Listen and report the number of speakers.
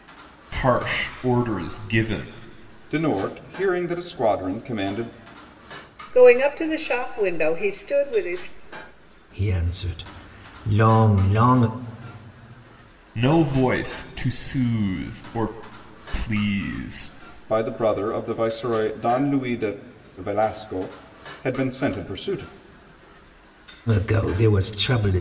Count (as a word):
four